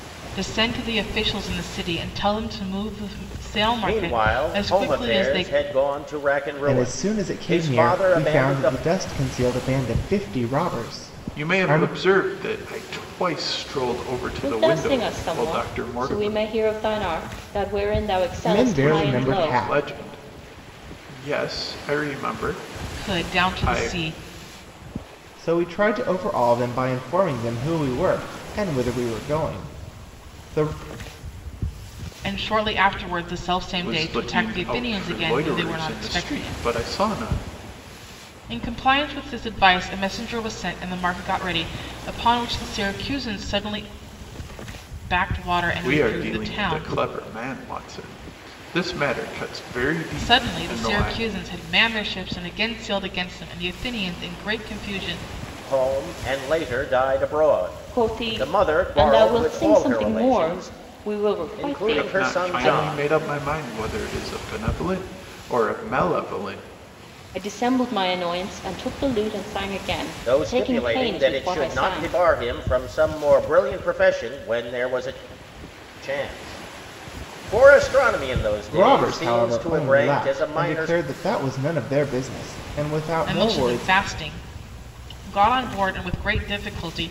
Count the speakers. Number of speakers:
5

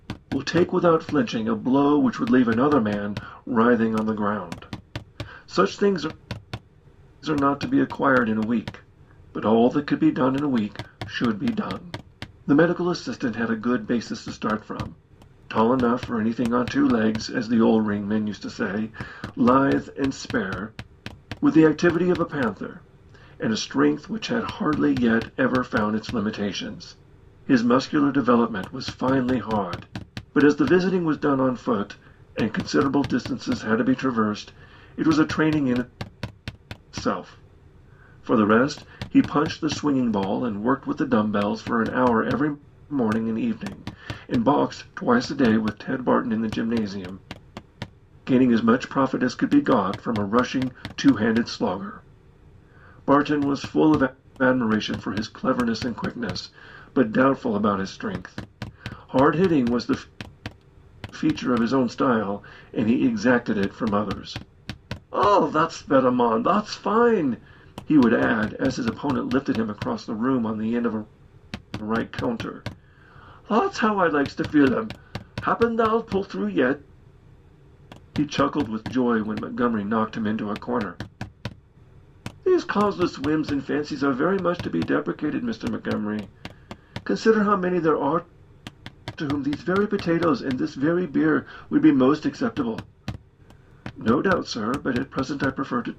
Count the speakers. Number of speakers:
1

